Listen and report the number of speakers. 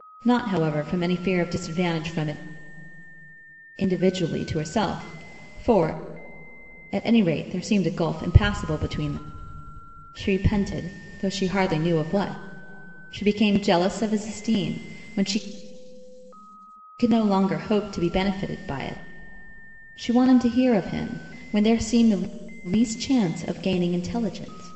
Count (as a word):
one